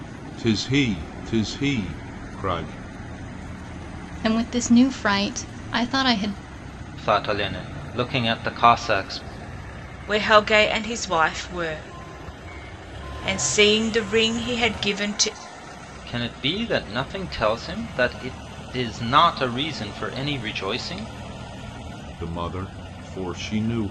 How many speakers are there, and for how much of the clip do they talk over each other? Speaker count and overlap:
four, no overlap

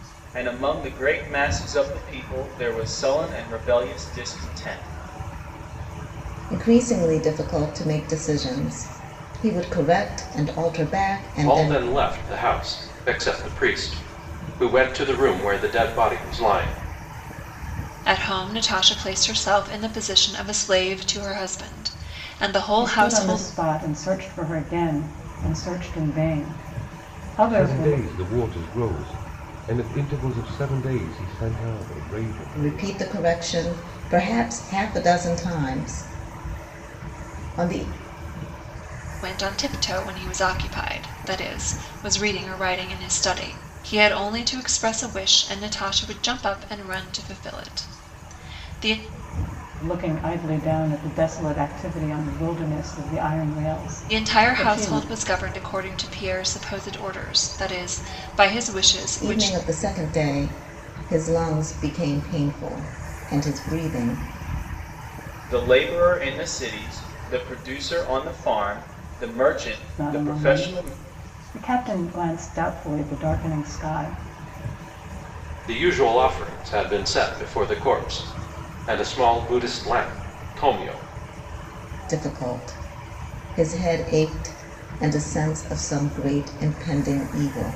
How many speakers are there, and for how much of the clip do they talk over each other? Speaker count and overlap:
six, about 5%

